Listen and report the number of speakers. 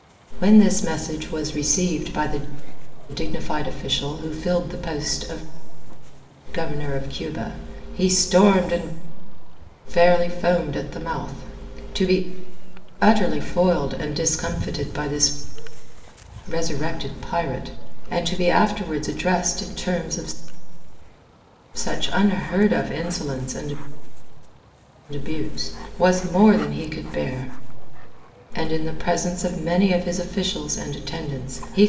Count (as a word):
one